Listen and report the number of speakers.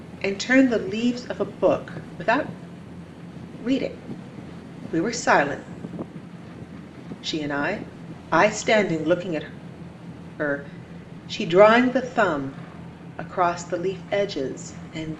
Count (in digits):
1